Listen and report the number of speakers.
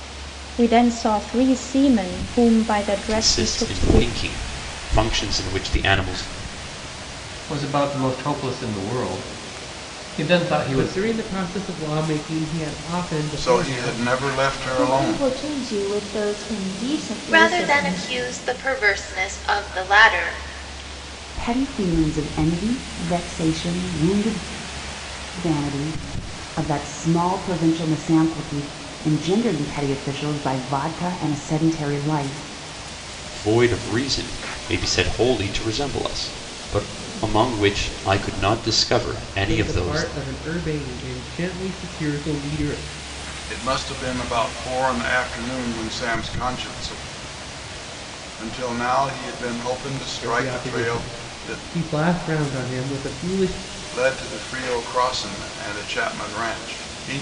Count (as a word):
eight